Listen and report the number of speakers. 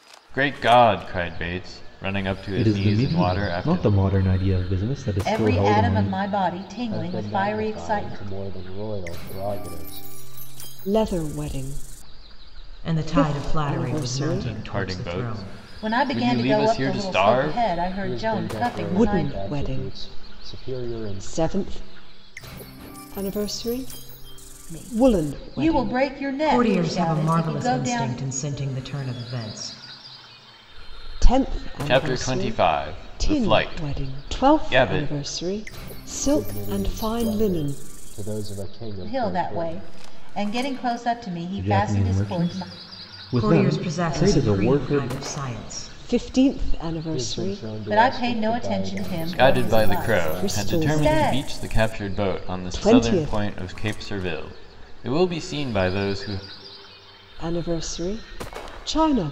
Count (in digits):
6